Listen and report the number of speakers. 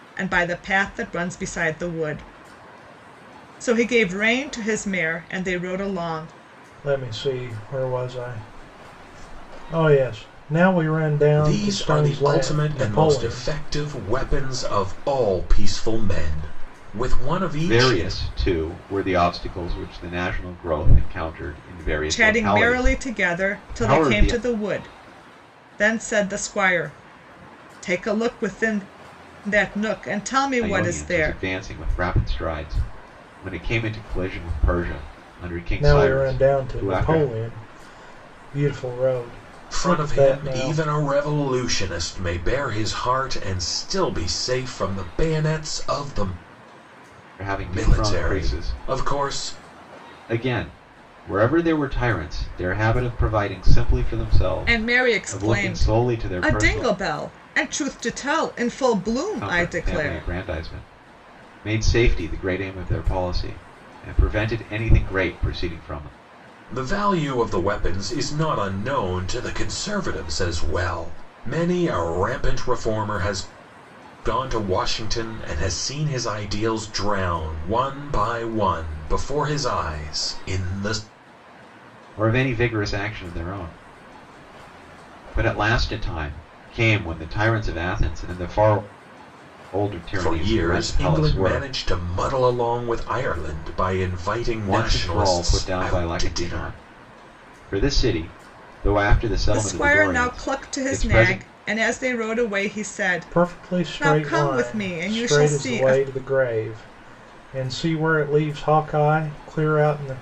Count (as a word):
four